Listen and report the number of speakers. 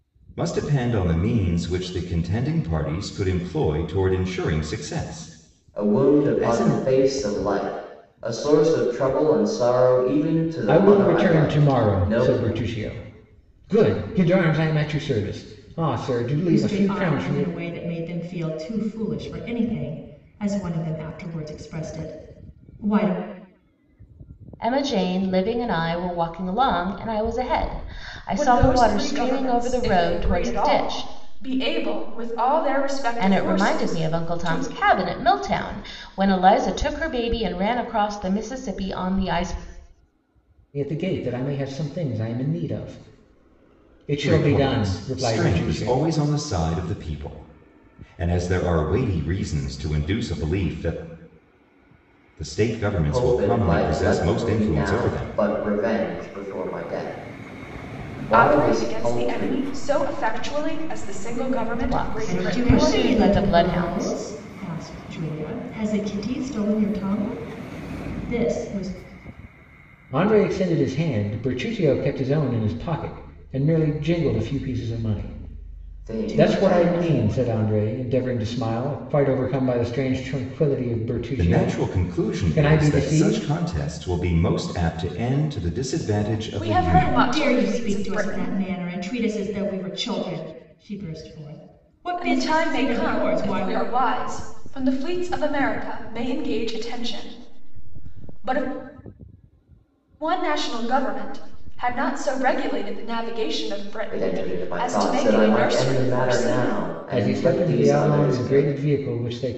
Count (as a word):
six